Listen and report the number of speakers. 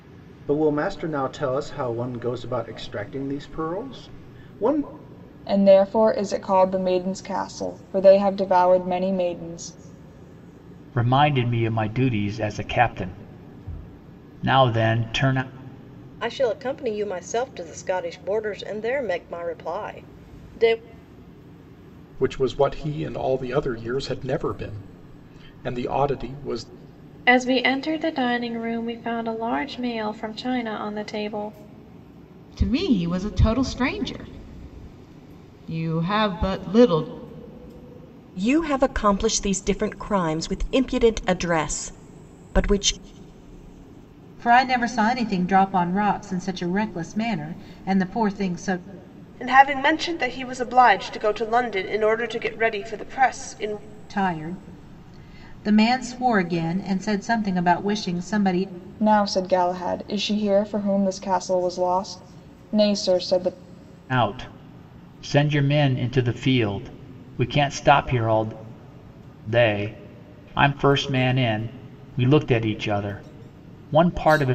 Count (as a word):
ten